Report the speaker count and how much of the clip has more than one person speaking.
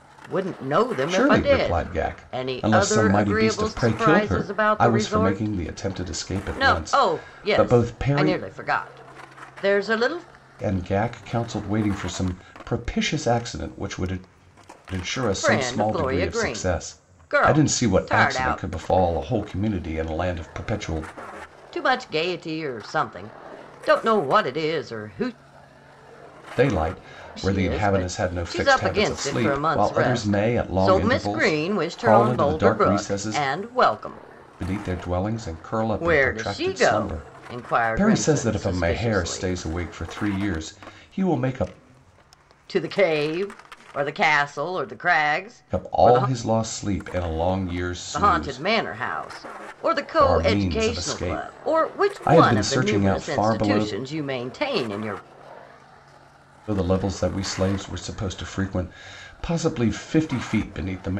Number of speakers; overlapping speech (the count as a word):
two, about 39%